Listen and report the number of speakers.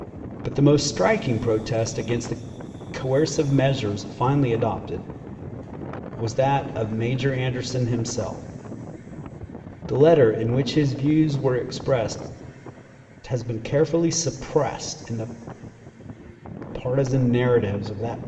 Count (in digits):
1